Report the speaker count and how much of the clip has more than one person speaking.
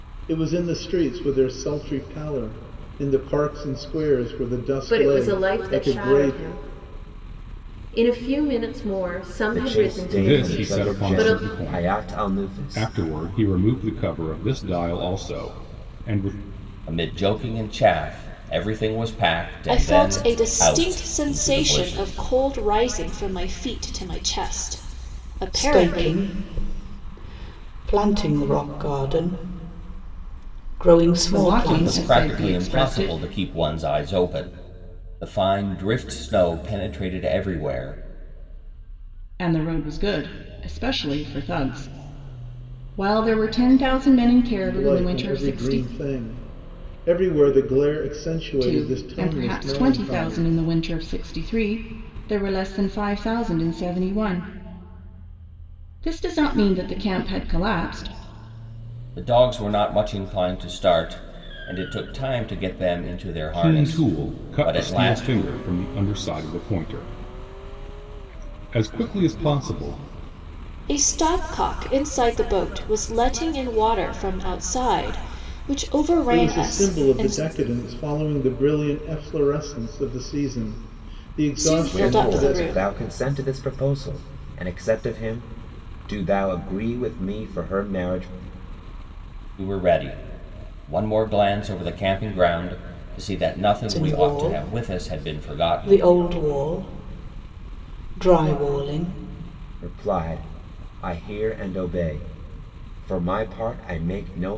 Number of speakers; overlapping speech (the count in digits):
8, about 19%